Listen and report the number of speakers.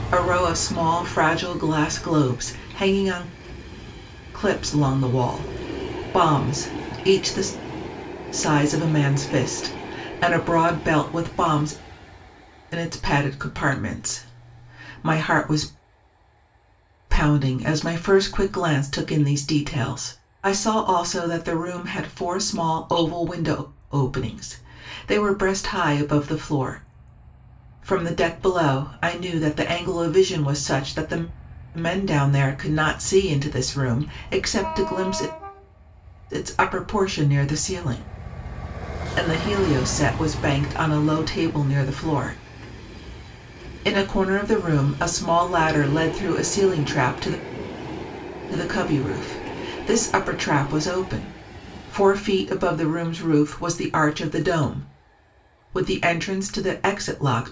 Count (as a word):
one